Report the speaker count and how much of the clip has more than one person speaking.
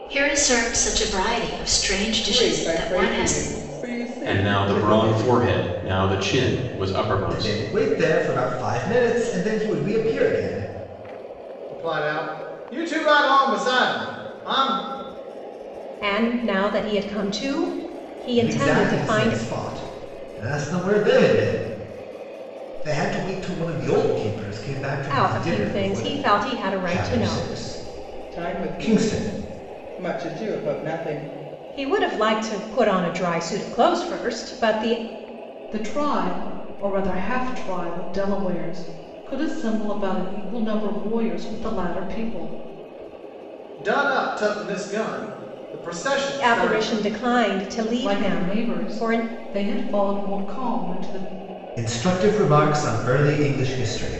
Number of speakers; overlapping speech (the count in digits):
6, about 15%